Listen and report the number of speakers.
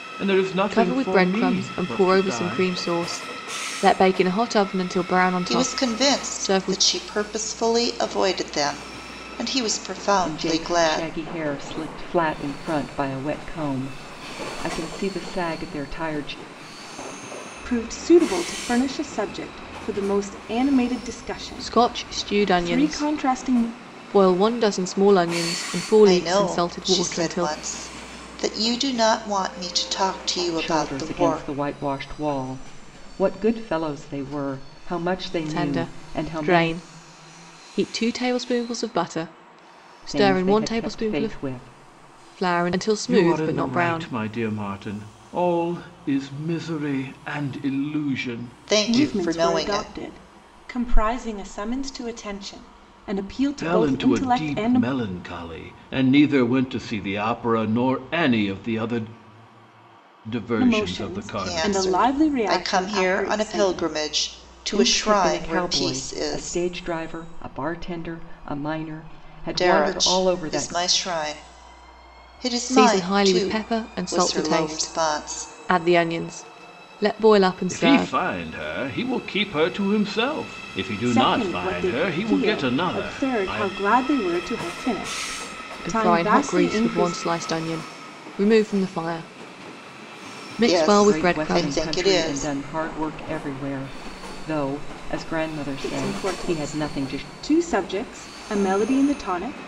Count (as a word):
five